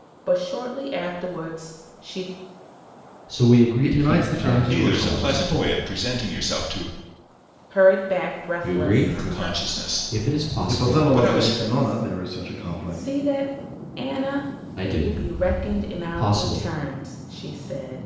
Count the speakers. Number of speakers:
4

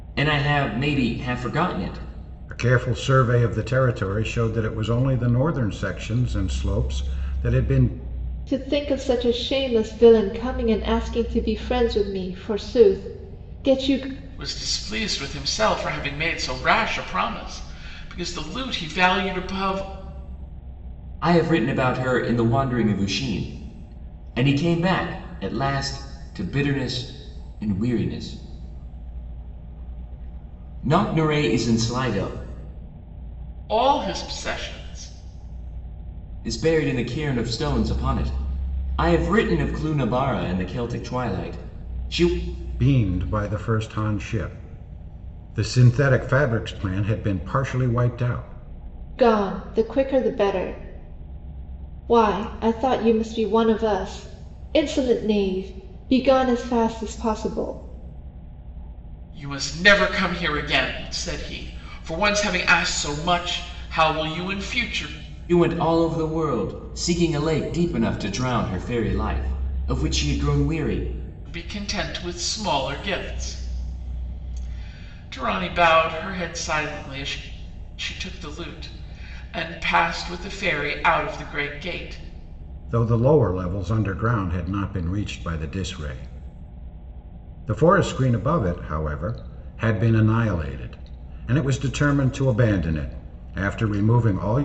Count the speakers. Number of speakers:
4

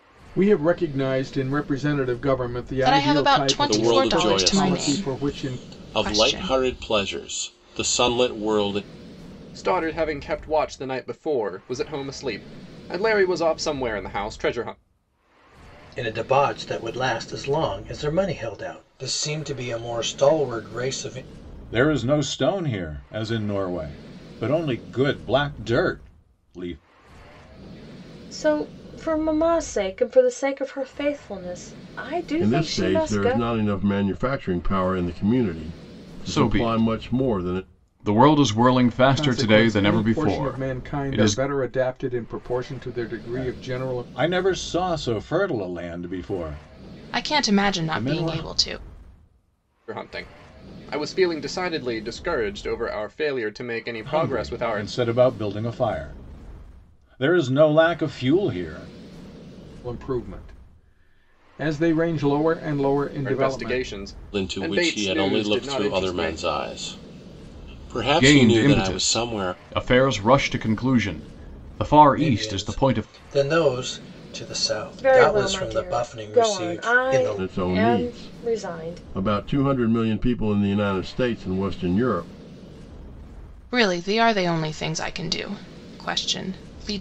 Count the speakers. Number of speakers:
9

